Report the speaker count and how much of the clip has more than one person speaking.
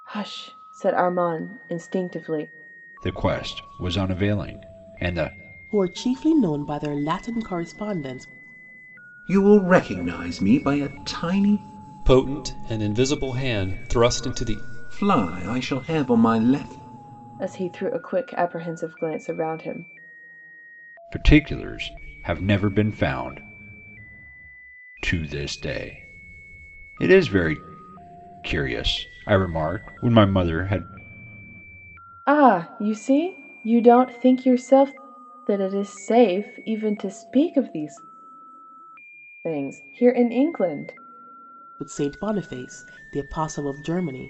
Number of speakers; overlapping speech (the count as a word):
five, no overlap